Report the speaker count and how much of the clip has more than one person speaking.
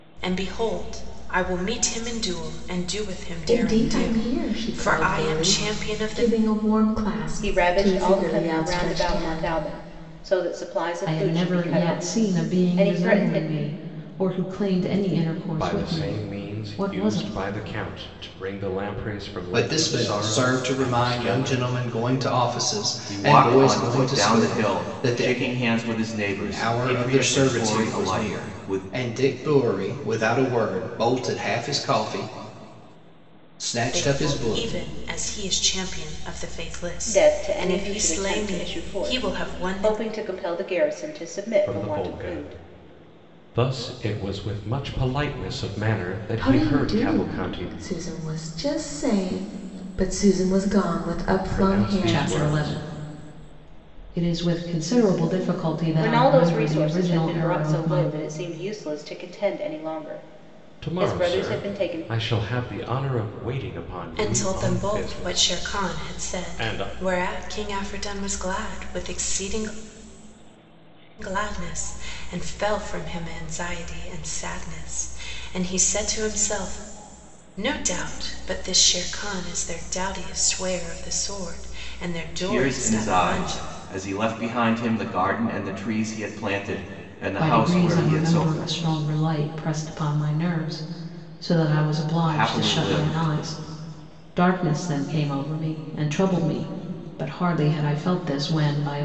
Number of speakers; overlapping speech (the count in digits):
7, about 34%